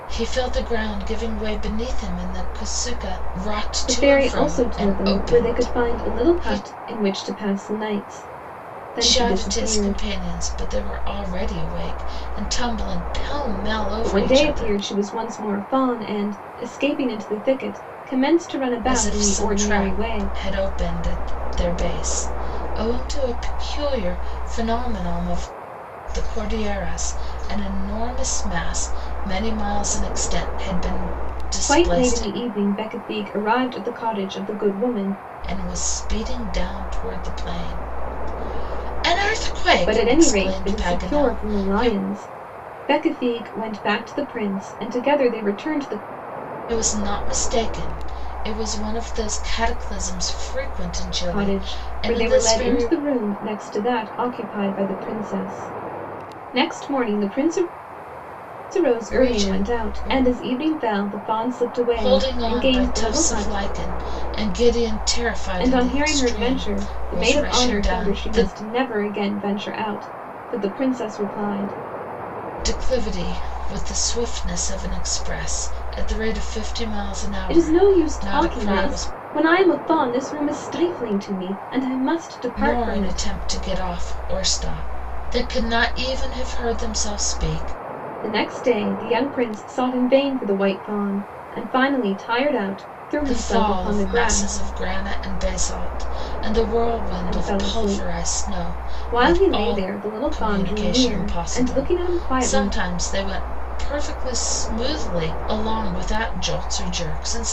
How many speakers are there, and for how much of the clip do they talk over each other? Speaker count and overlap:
two, about 24%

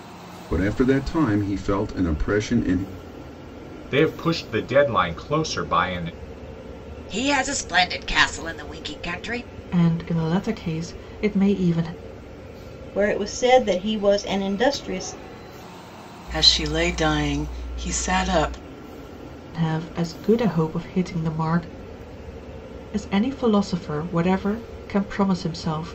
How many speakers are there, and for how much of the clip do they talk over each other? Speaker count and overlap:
six, no overlap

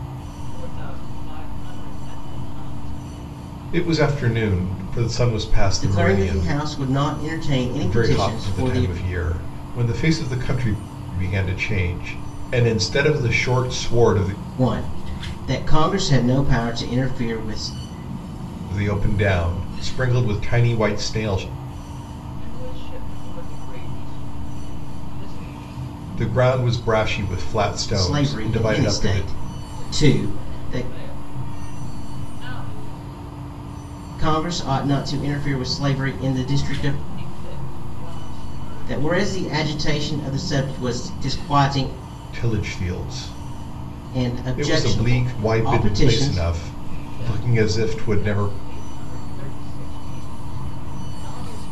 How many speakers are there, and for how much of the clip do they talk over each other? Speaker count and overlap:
three, about 18%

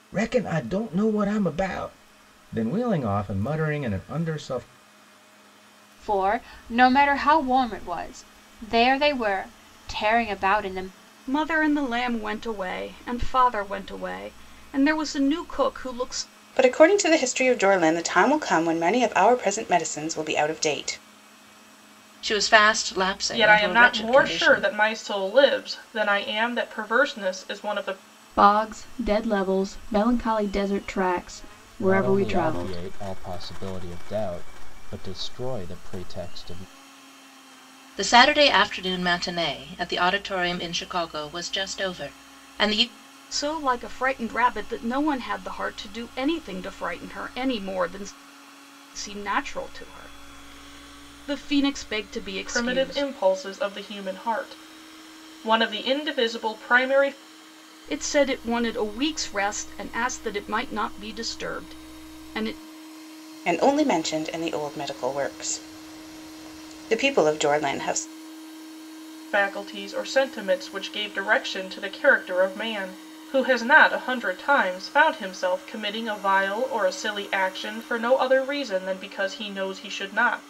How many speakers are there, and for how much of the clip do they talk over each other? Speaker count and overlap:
eight, about 4%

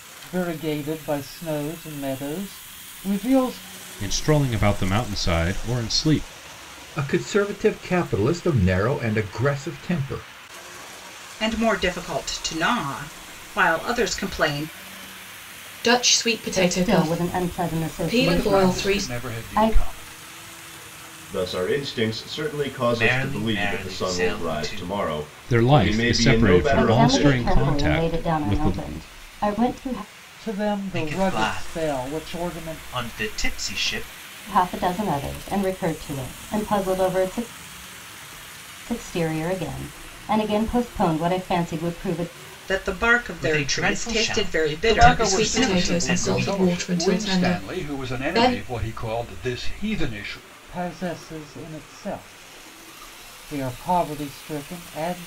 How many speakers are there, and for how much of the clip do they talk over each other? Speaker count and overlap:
nine, about 29%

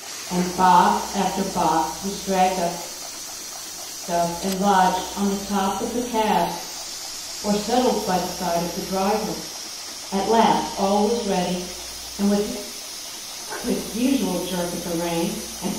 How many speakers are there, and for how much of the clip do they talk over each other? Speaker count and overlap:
one, no overlap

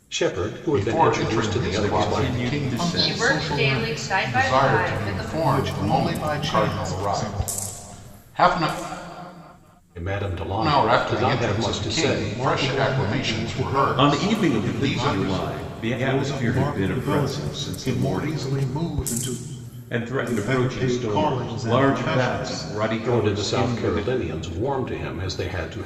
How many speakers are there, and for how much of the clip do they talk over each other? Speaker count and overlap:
five, about 70%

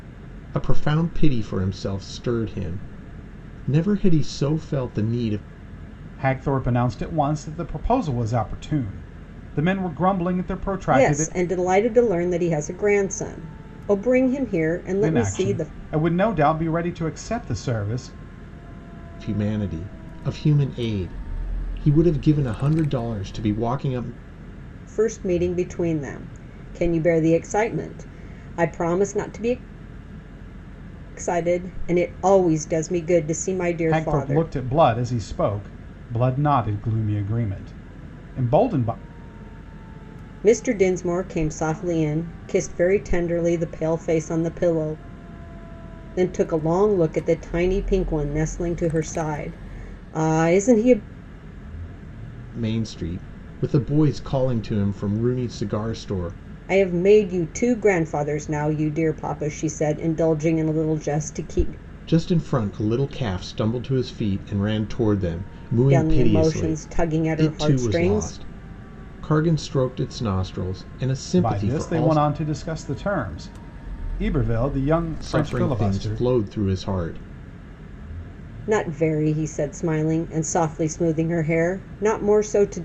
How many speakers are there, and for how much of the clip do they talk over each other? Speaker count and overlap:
three, about 7%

